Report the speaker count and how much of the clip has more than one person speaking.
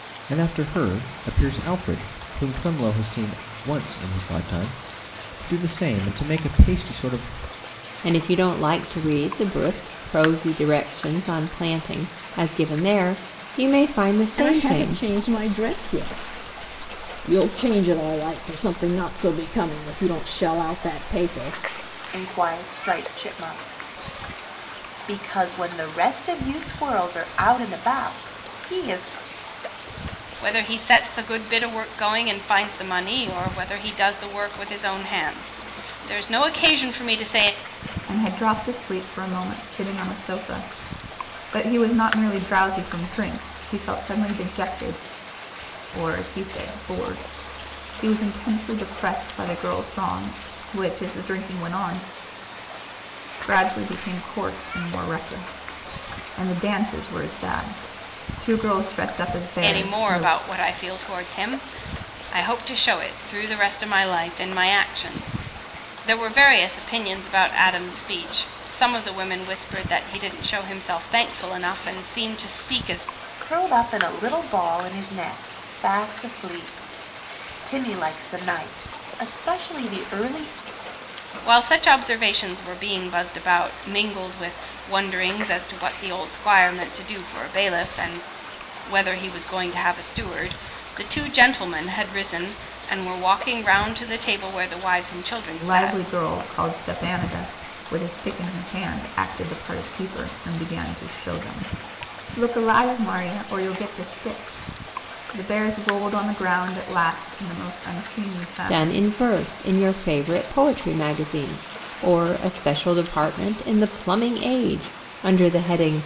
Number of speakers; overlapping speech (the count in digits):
6, about 2%